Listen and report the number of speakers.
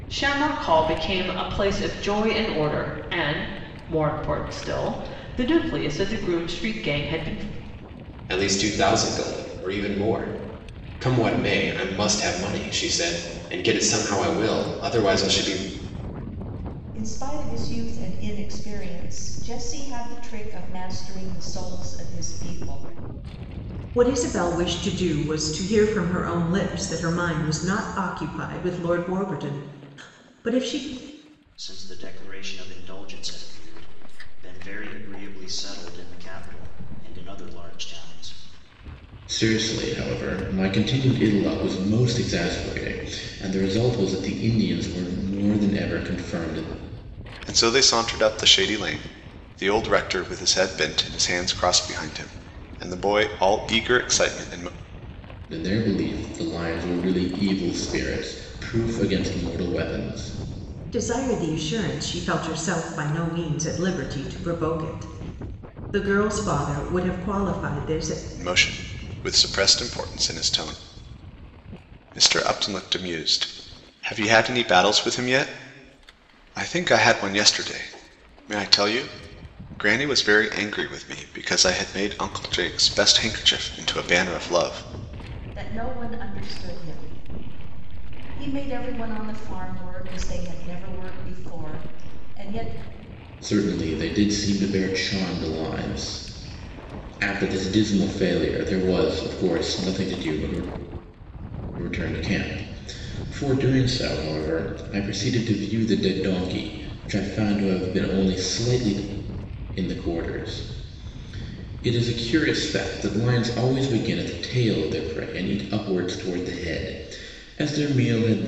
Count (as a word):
seven